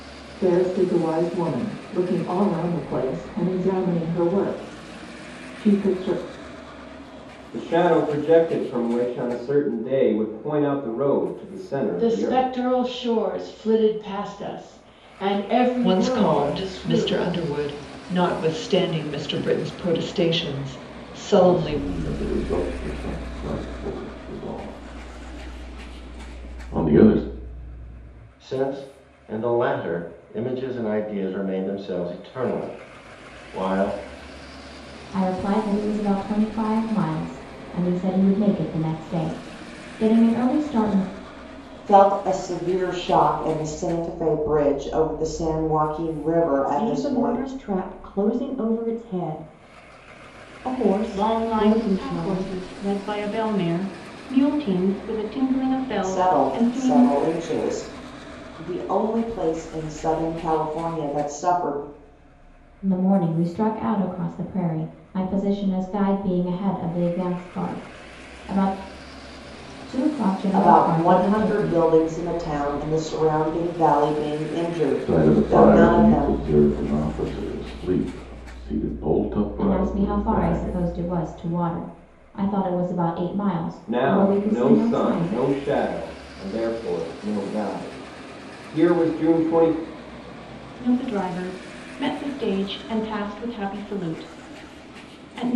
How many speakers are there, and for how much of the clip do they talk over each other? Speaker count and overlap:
10, about 12%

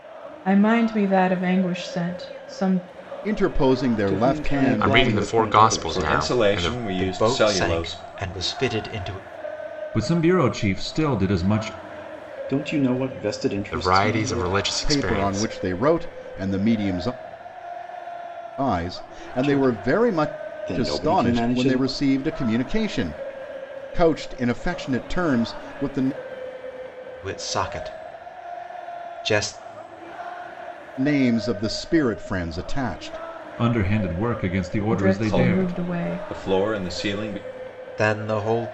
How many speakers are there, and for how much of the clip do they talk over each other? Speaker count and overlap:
7, about 23%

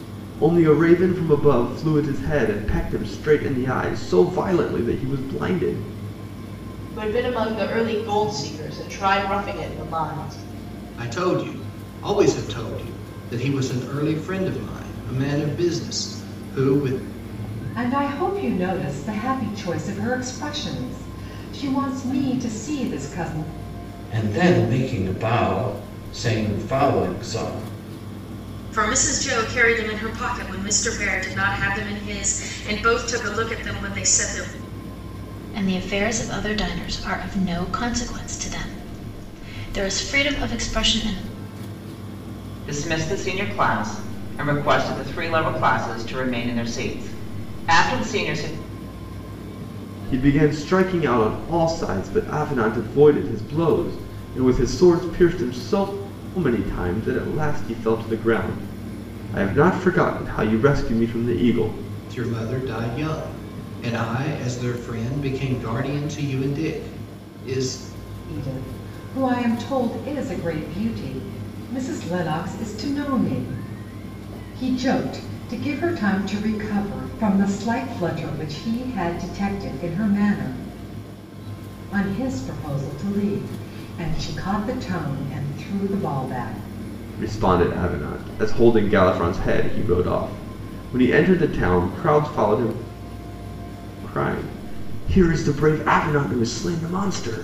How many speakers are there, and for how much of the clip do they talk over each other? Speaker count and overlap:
8, no overlap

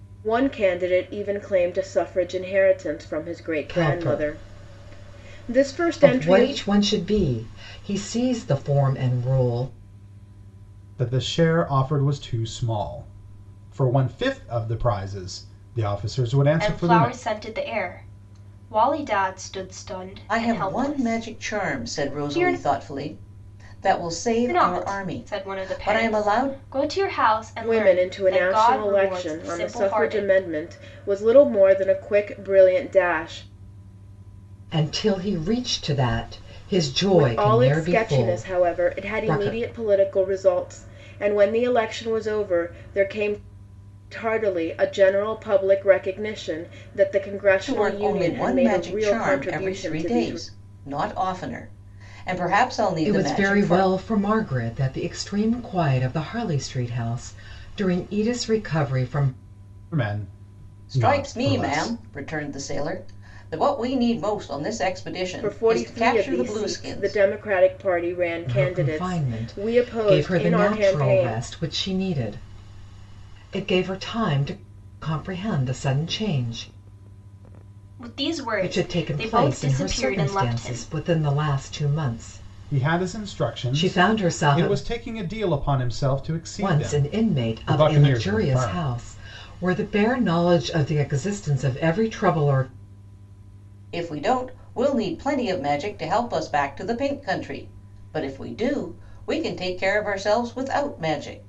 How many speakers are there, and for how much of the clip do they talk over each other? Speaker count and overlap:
5, about 29%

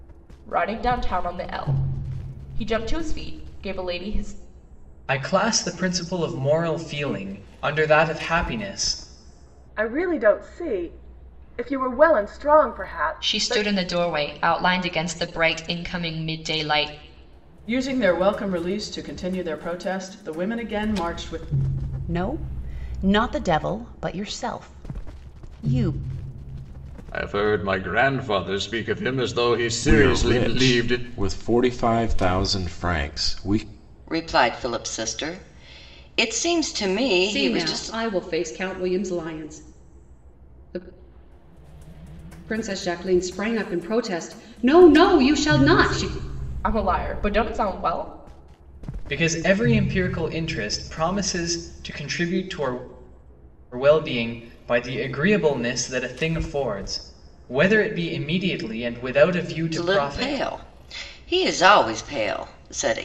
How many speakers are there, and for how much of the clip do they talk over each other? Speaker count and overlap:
10, about 5%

